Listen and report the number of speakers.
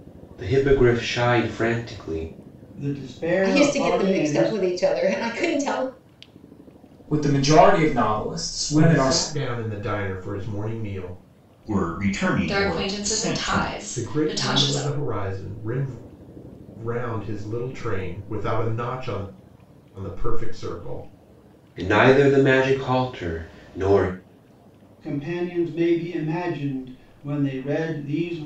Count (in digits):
7